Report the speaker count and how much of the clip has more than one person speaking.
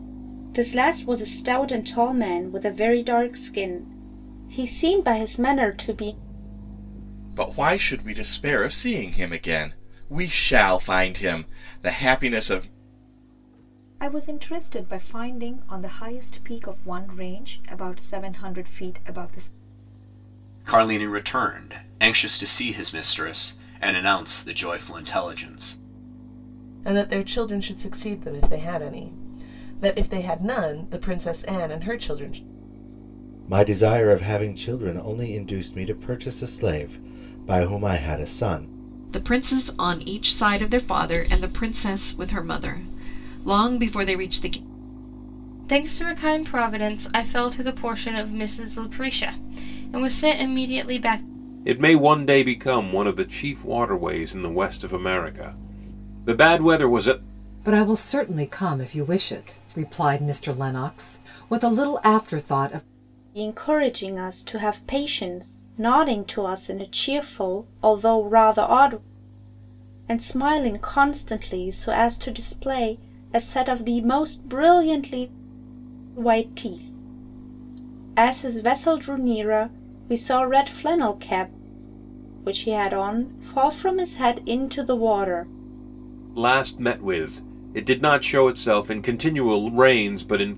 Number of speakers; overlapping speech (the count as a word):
ten, no overlap